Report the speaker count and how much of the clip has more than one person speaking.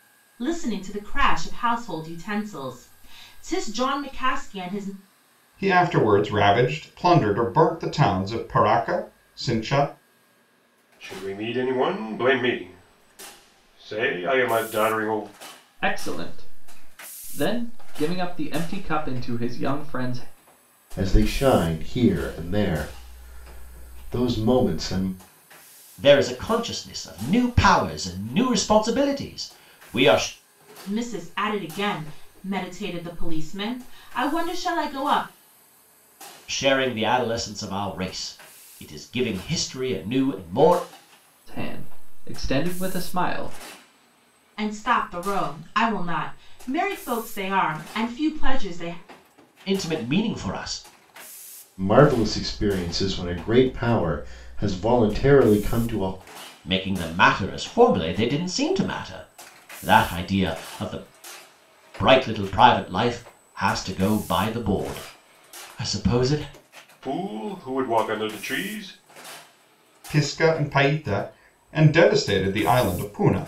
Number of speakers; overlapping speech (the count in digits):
6, no overlap